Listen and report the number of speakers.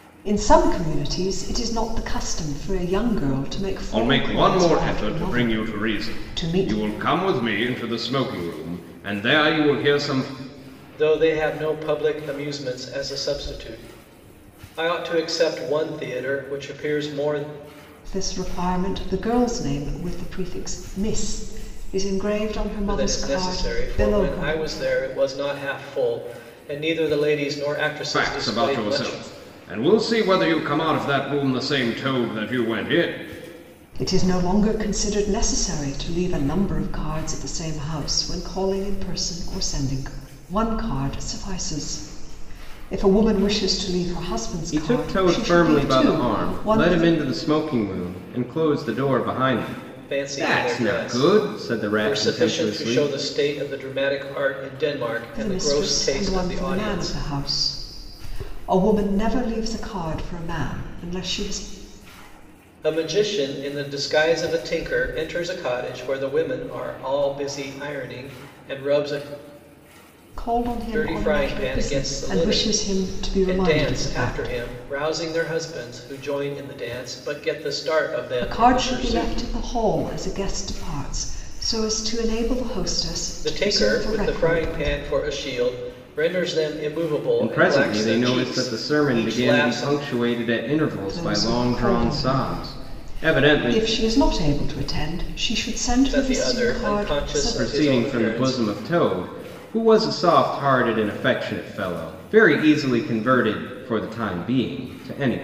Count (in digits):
3